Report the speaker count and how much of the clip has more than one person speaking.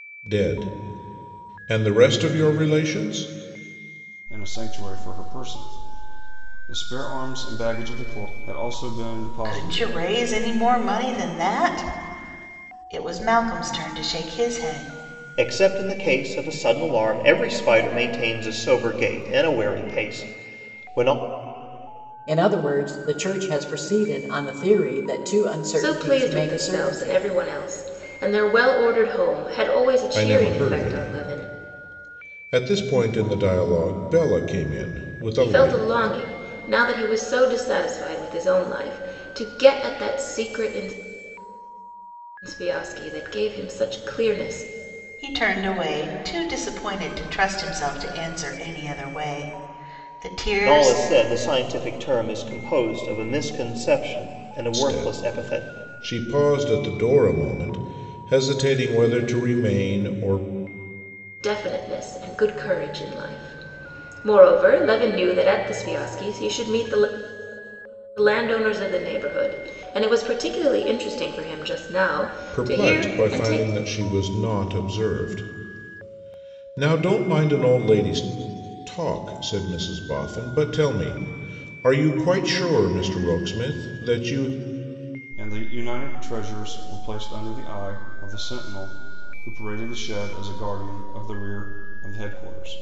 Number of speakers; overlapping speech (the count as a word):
six, about 7%